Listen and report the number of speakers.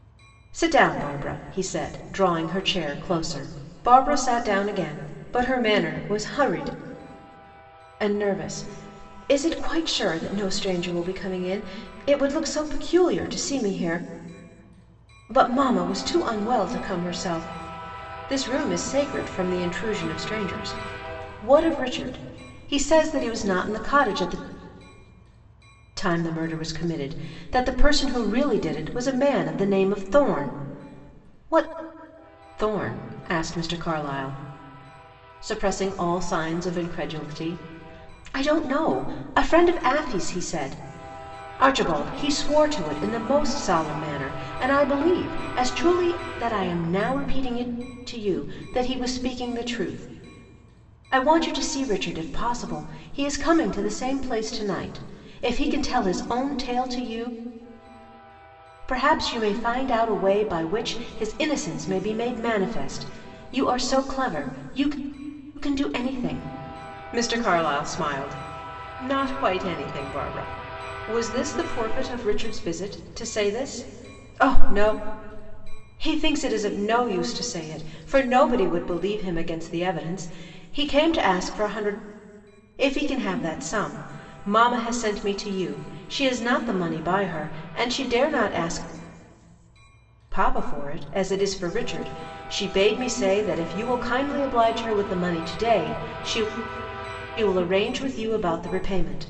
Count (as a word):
one